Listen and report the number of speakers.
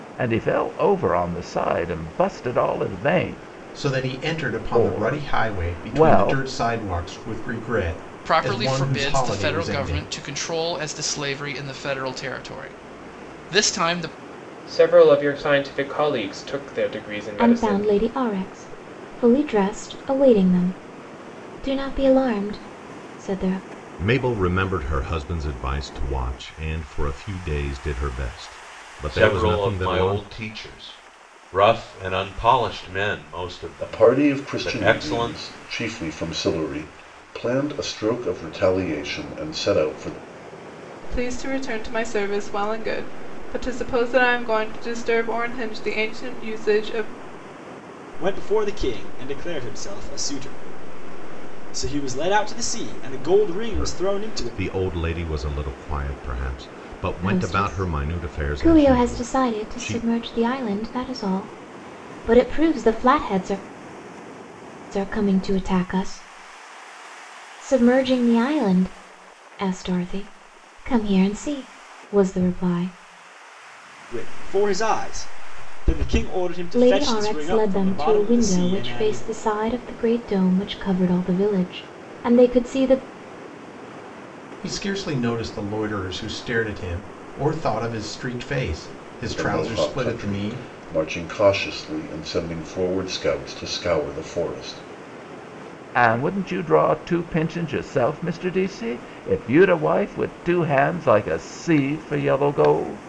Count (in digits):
10